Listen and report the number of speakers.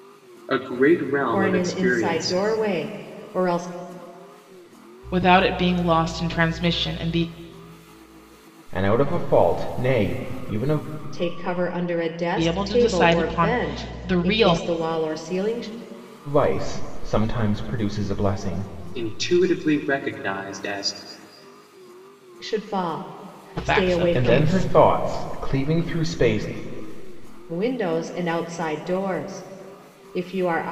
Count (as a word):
four